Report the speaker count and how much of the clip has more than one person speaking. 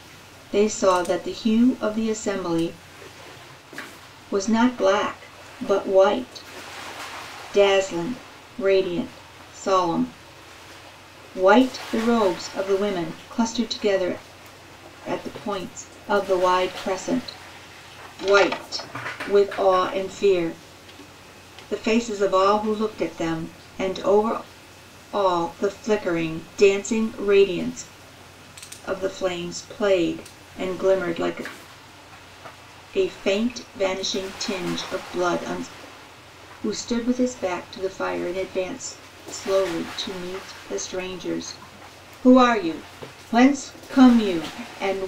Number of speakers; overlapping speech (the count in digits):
1, no overlap